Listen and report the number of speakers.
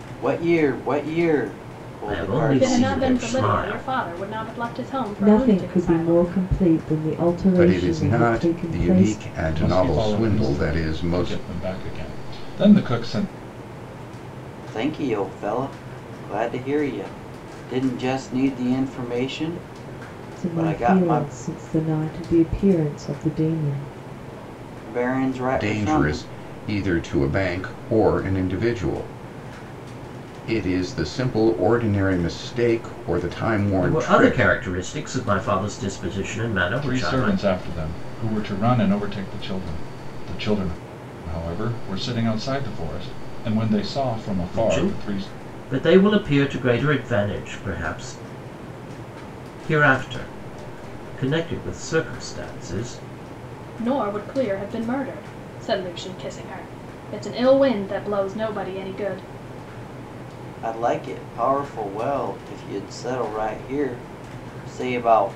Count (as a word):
six